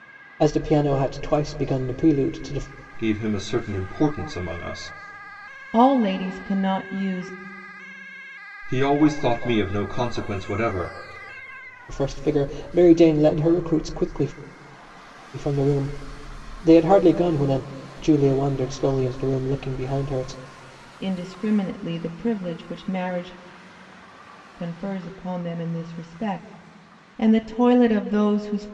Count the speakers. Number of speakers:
3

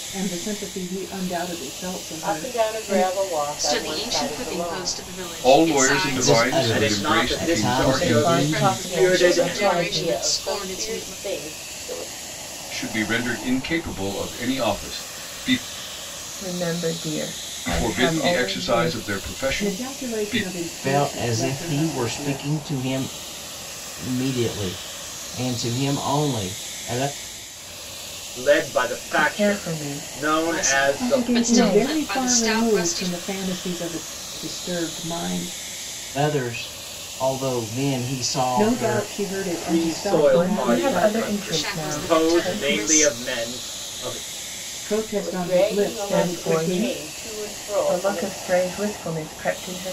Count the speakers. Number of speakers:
7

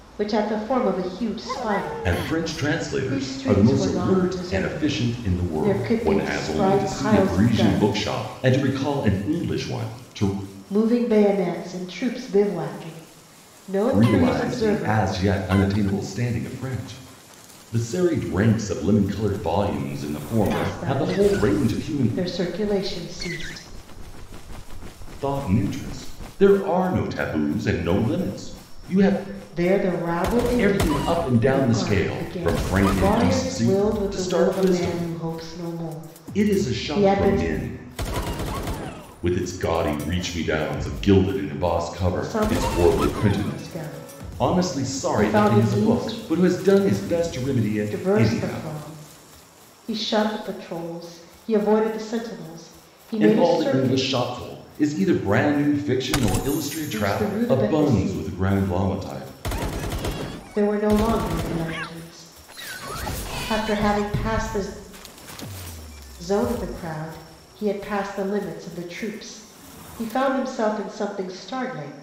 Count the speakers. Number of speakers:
2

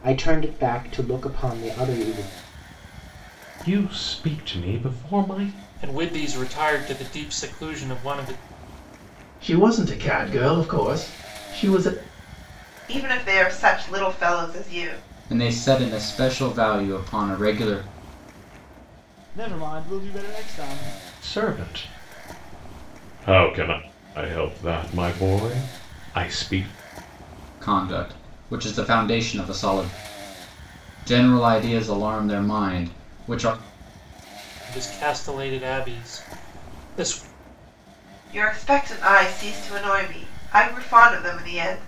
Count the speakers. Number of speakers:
7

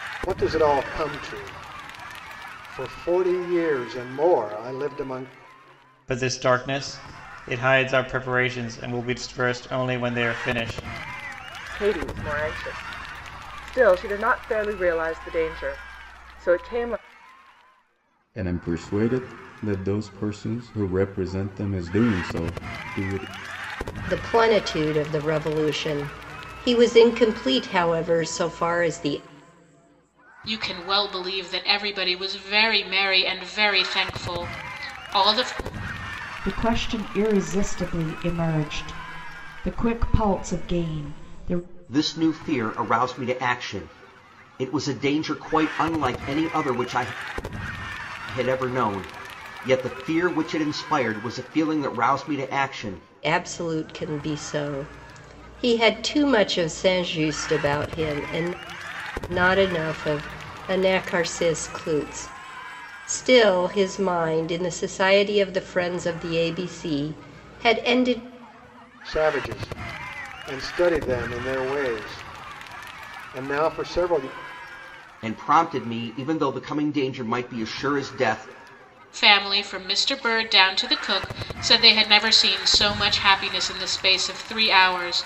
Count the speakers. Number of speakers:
8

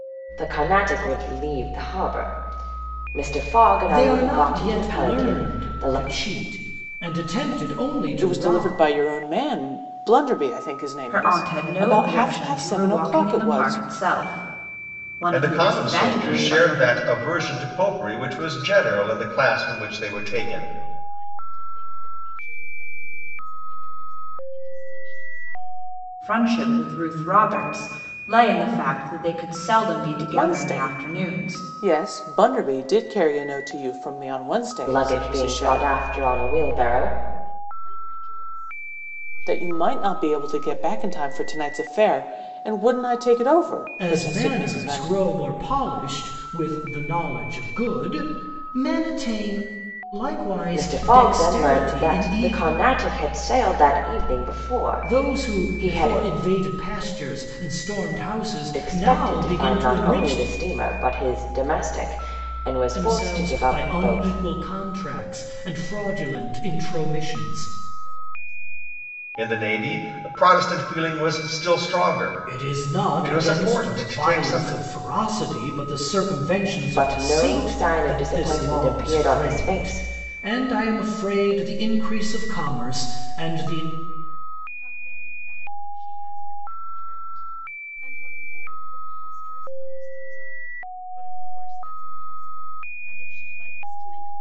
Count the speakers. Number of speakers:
6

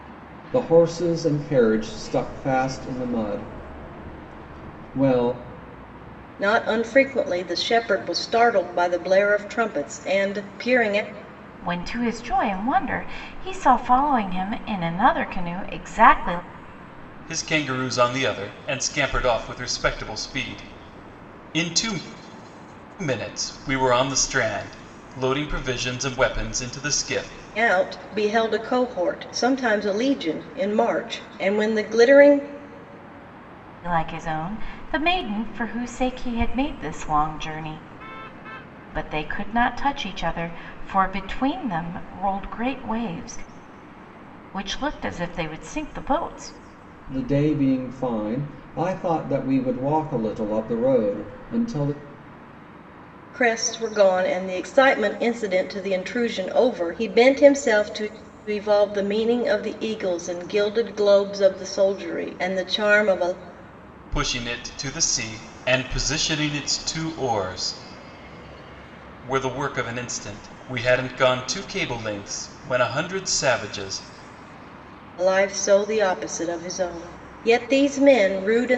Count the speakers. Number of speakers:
4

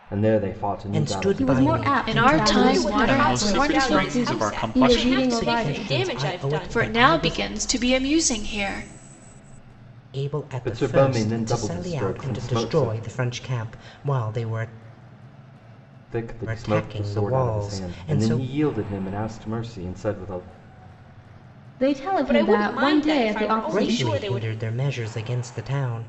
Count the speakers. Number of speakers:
6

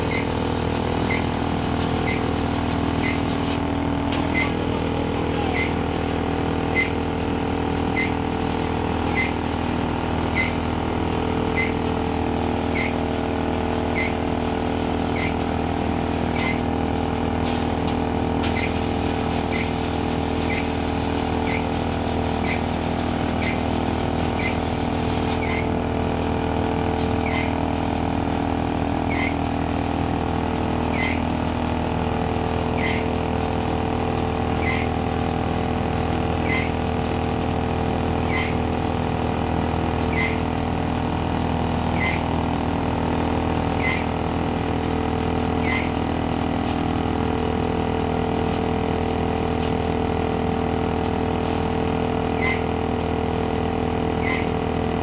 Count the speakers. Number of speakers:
0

